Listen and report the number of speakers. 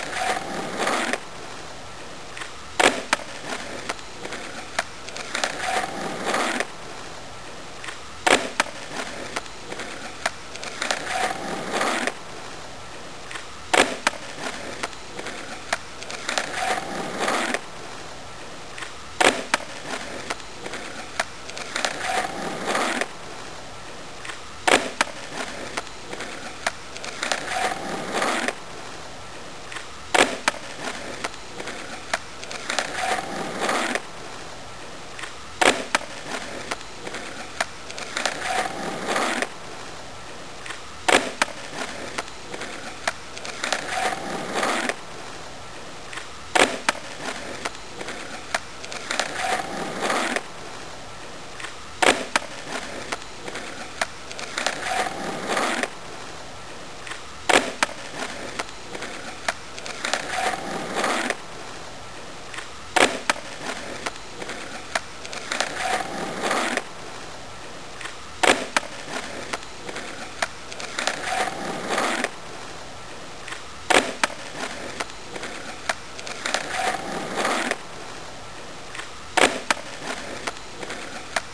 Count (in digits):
0